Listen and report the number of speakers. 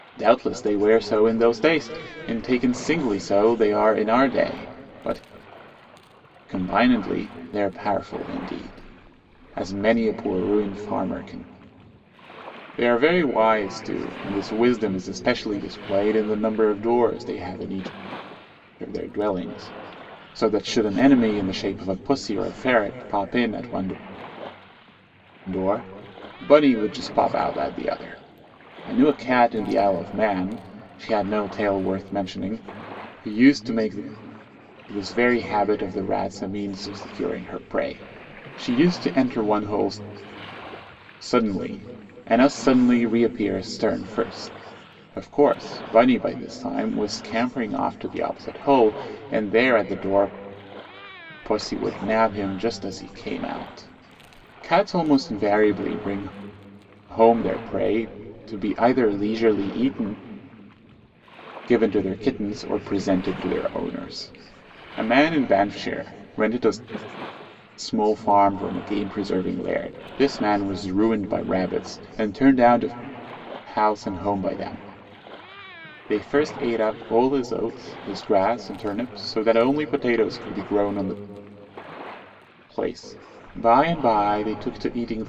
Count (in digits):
1